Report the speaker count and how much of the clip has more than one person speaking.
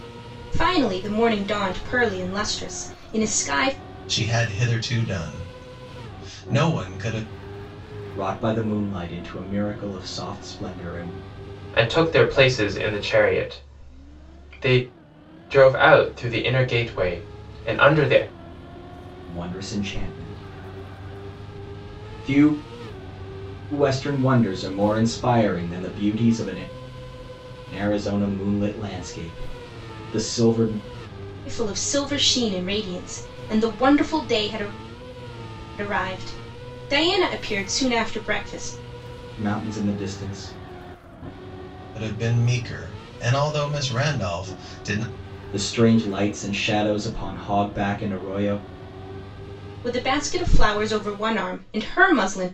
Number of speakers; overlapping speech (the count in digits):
4, no overlap